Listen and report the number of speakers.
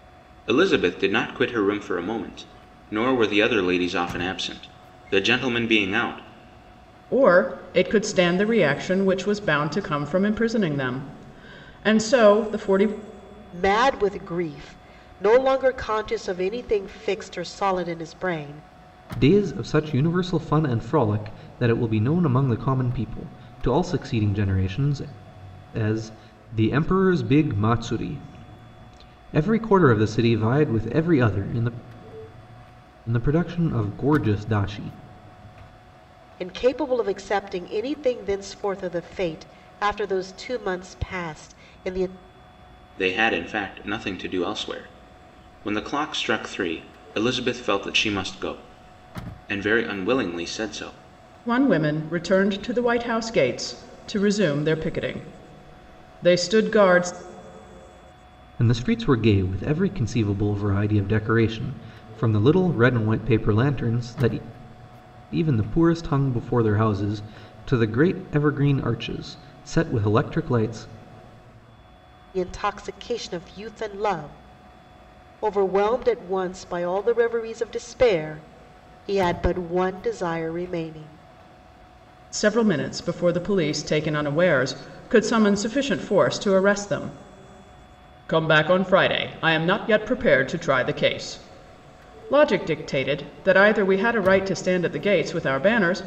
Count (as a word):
four